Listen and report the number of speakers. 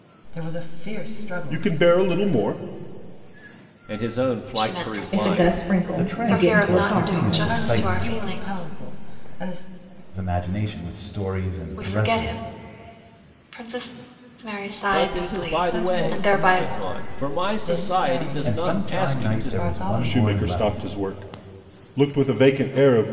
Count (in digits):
6